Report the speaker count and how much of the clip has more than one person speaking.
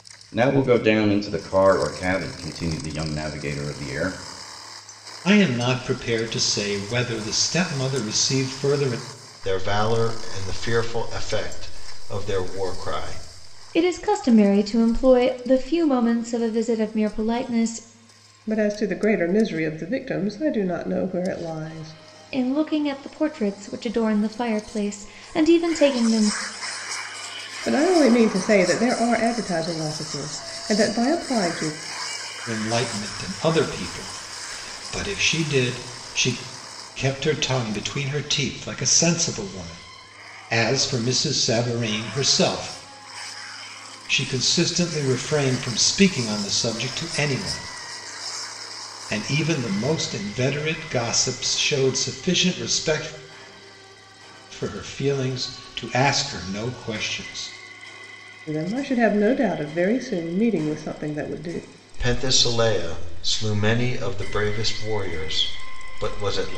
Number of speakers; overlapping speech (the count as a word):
five, no overlap